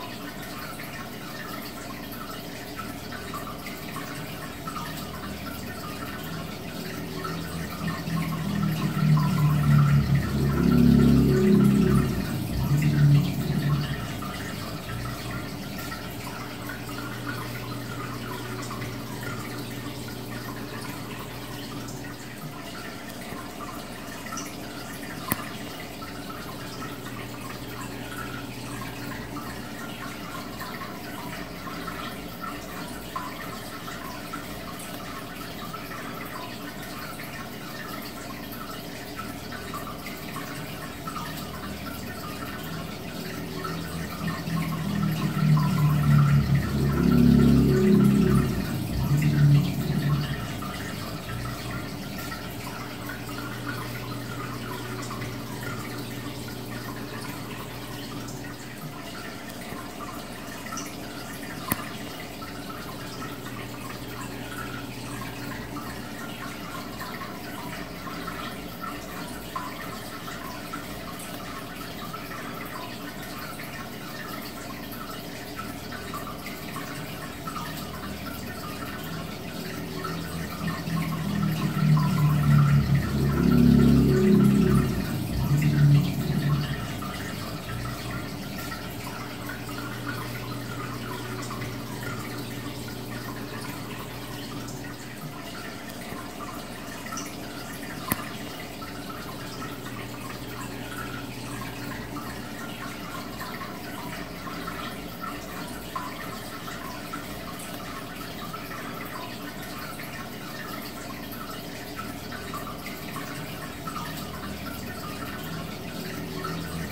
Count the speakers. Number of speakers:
0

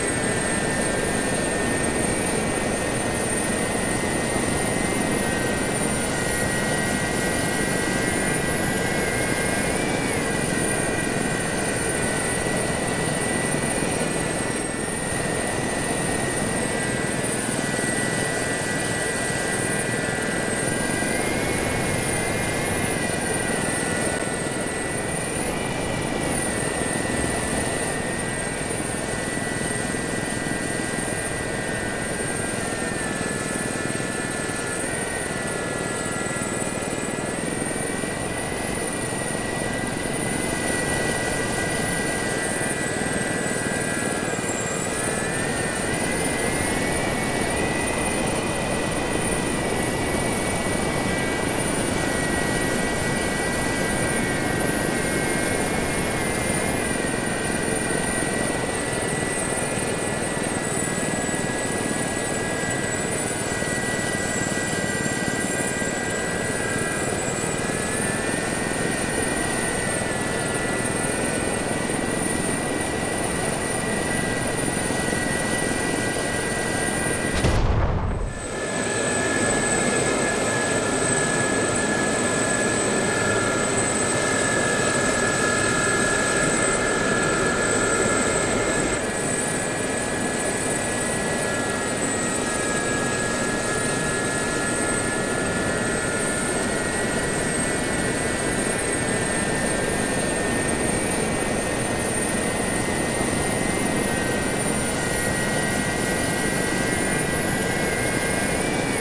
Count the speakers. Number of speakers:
0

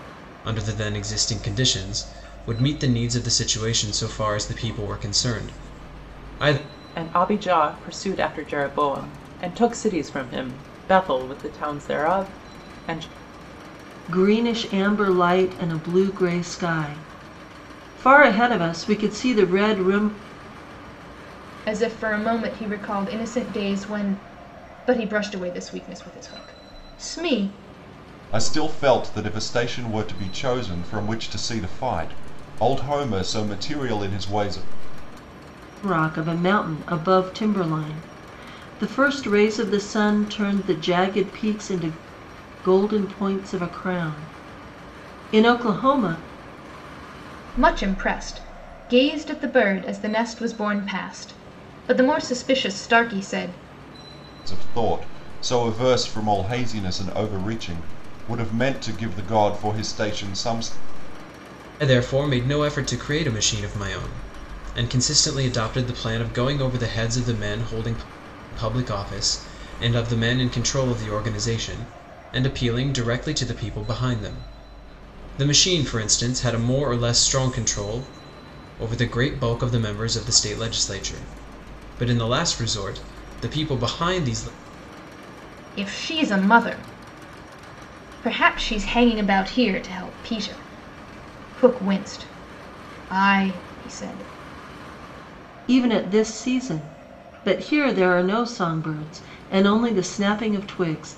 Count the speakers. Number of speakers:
5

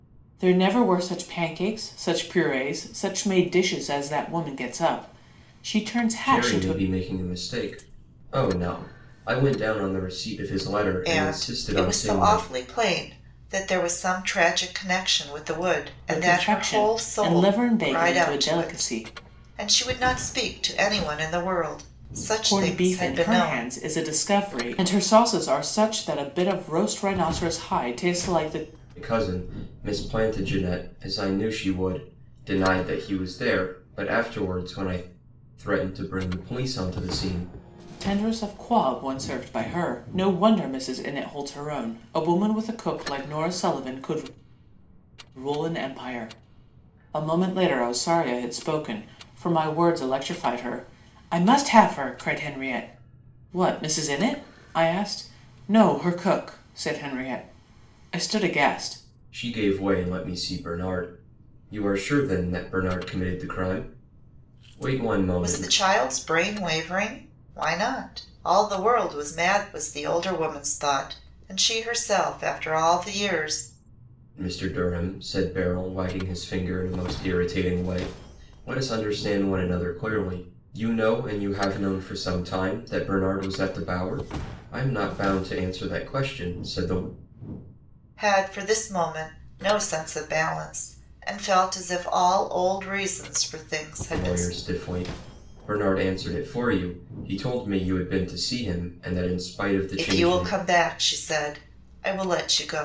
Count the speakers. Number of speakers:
3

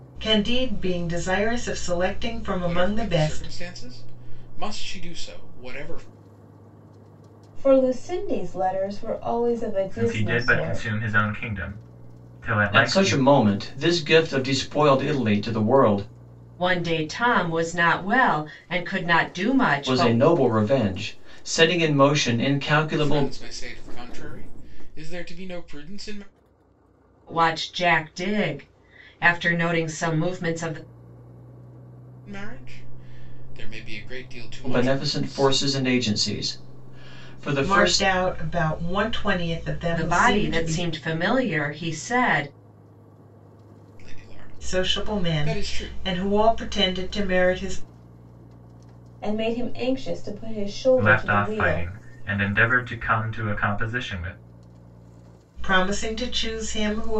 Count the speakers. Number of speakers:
6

